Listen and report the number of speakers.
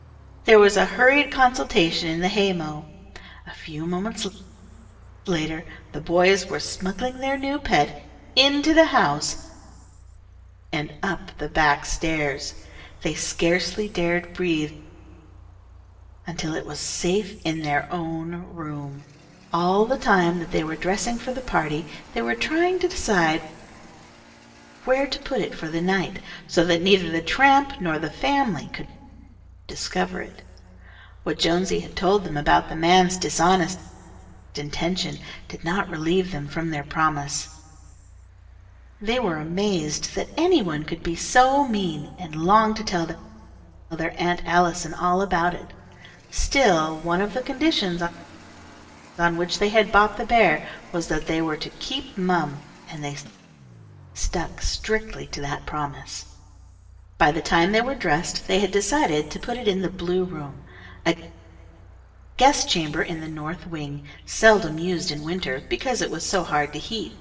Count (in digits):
1